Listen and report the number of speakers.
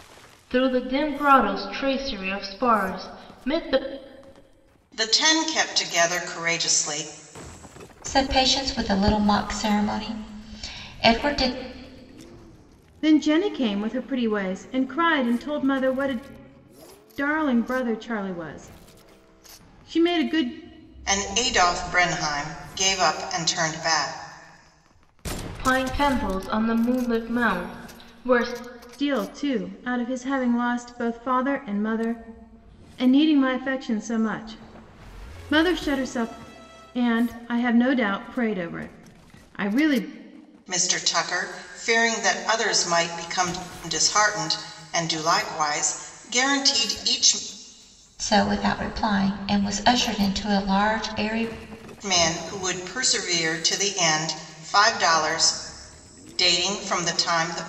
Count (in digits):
4